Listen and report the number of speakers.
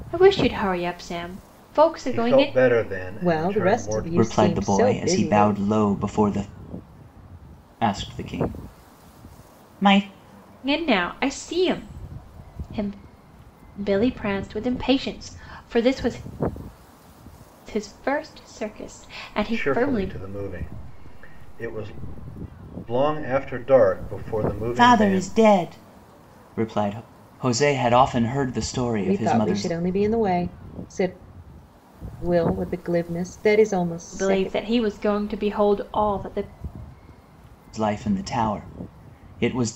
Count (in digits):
4